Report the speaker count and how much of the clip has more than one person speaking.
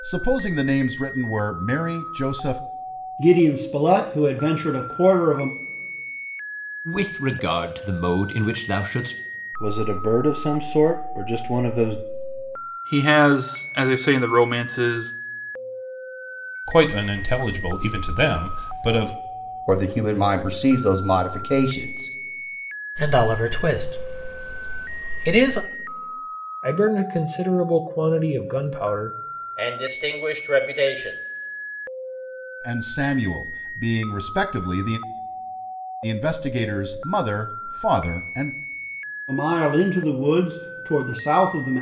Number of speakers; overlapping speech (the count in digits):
10, no overlap